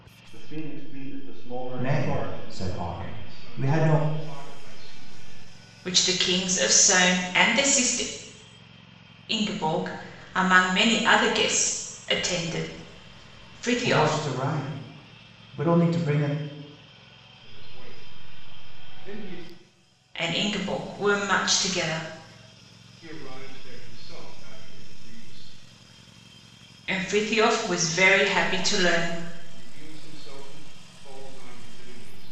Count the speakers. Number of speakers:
four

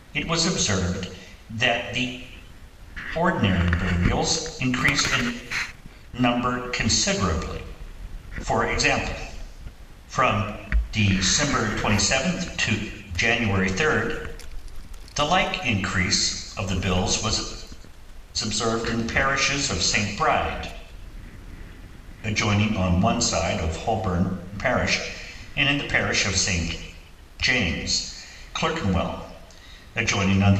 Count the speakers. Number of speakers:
one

